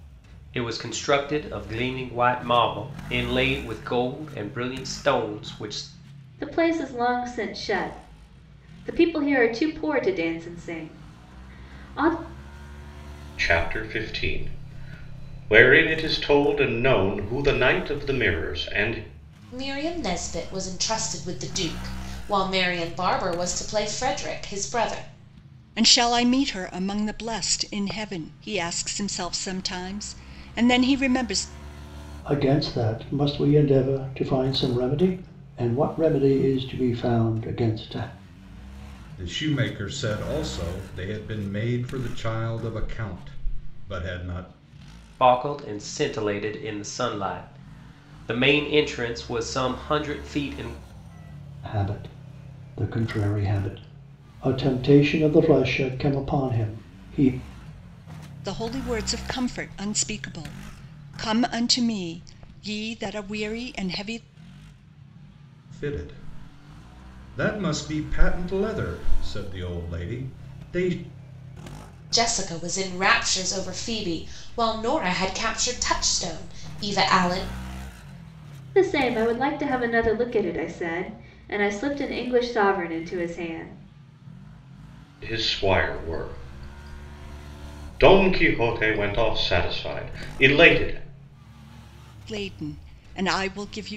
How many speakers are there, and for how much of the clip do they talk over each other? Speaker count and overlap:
seven, no overlap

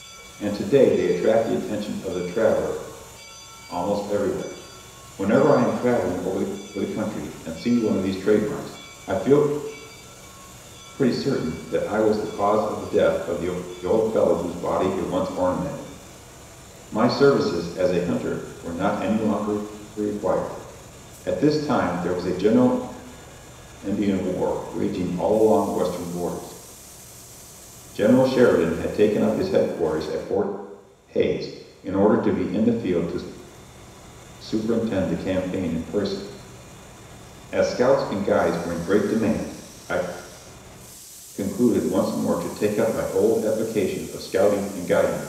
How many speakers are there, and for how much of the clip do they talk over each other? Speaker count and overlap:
one, no overlap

